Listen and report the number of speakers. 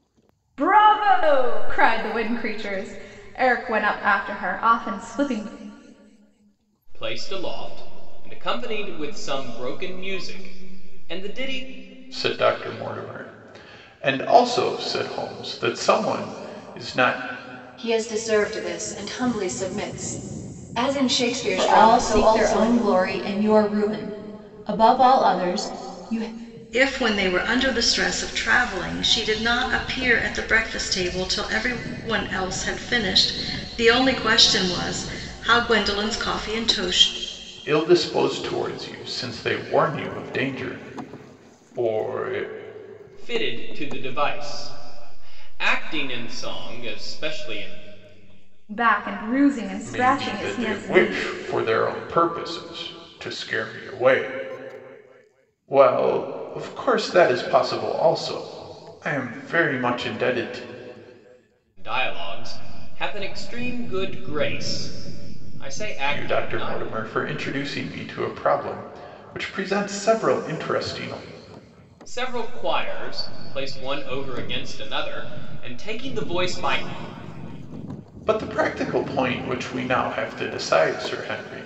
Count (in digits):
6